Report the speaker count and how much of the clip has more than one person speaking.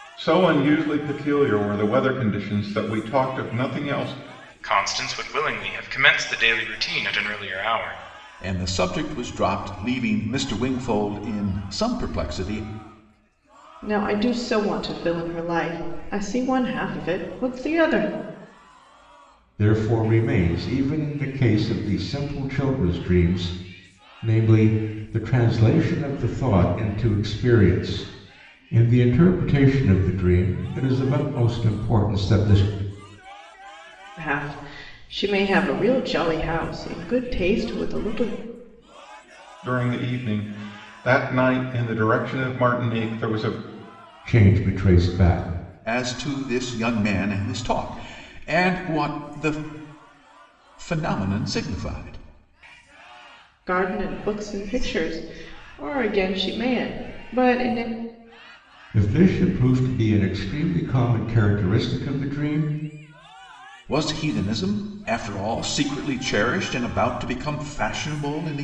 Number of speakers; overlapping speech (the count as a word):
five, no overlap